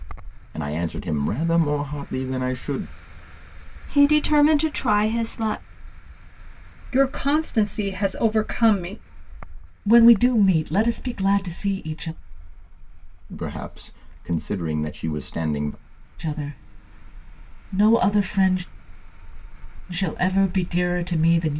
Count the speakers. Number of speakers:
4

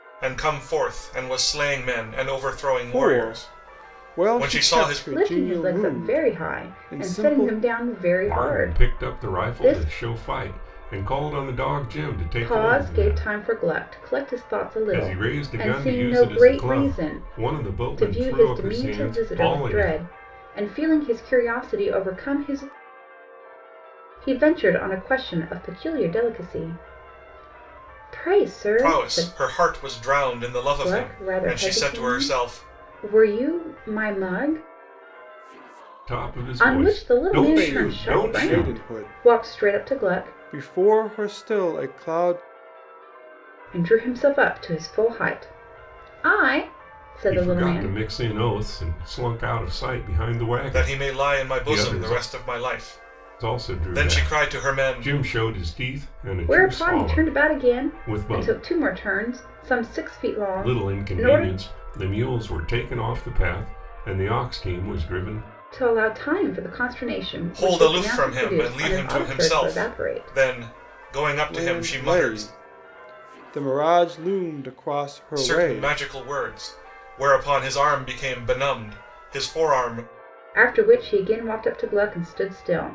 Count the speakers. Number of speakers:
4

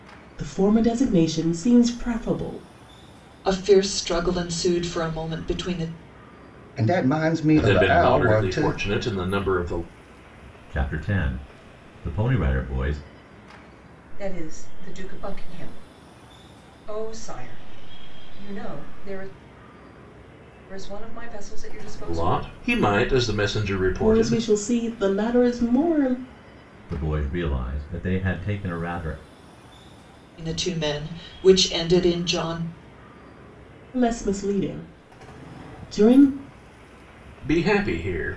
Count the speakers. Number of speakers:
6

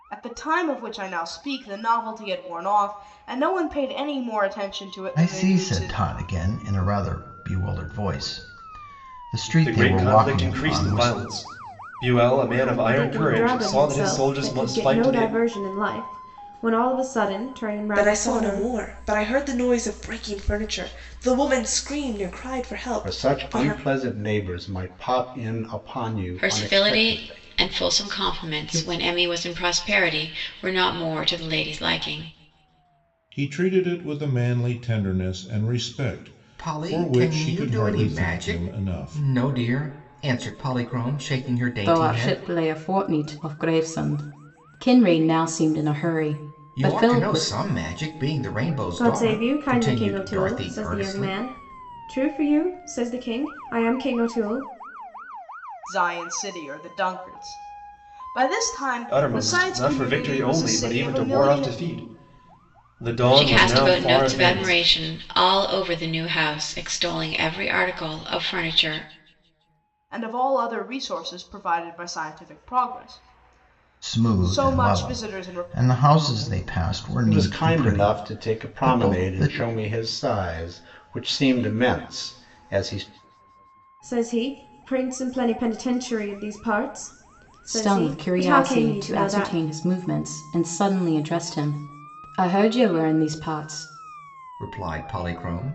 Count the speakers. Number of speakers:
10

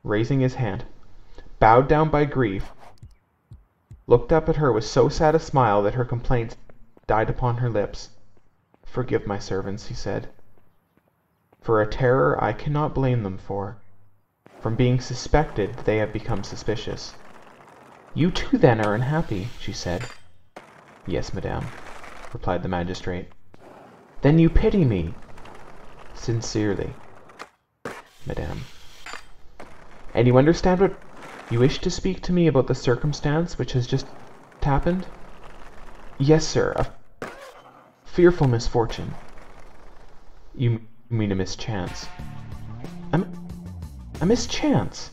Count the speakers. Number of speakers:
1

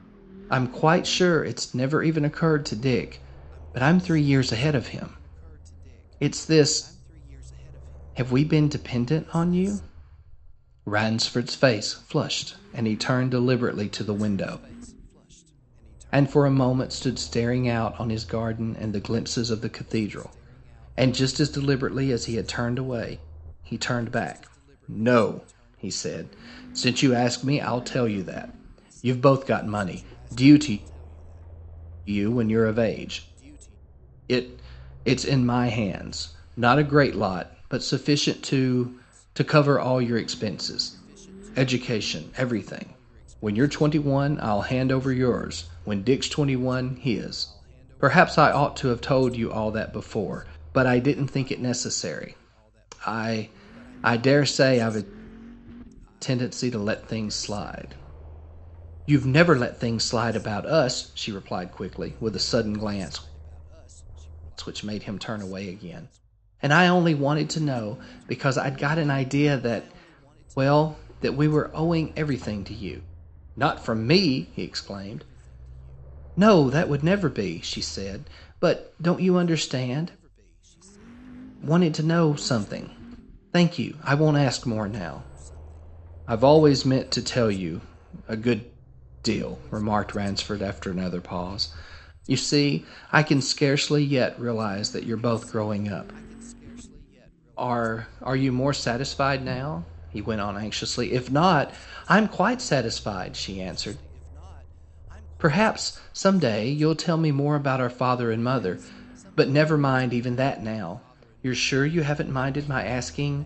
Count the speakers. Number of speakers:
1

